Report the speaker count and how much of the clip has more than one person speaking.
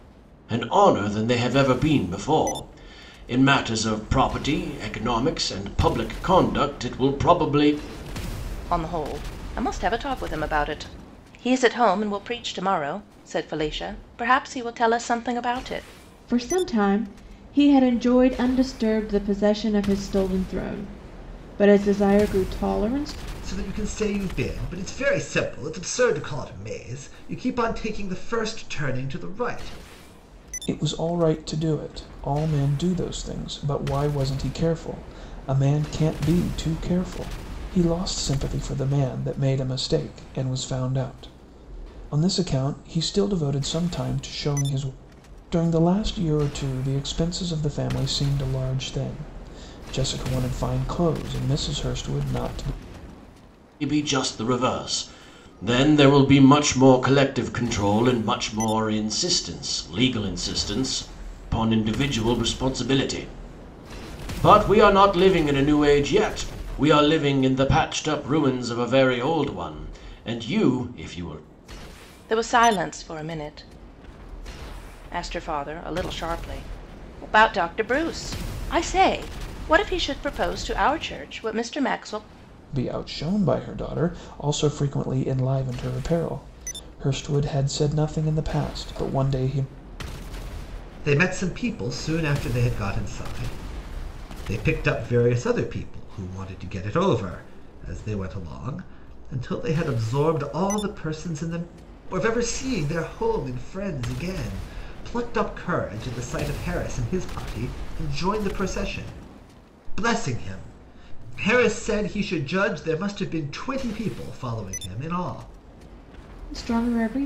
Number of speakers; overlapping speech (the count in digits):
5, no overlap